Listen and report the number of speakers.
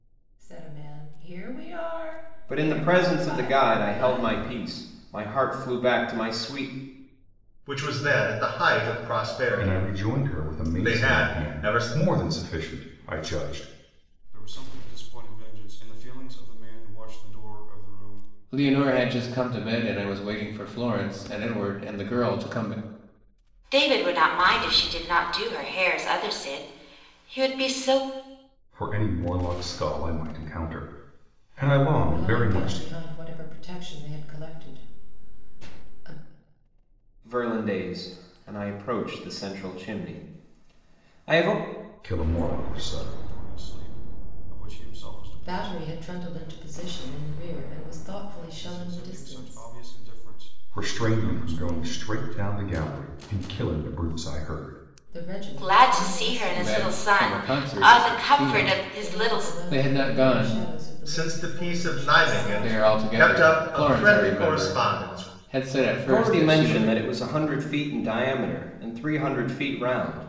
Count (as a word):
seven